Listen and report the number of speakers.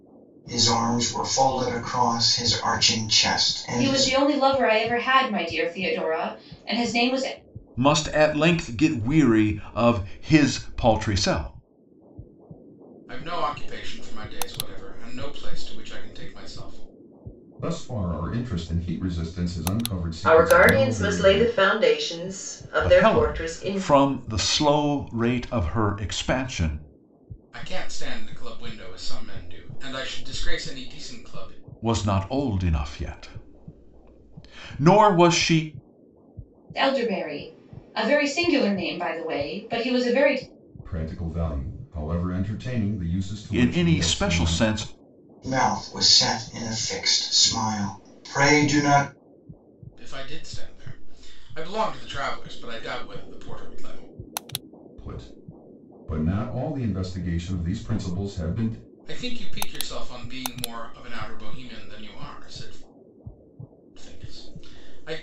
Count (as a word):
six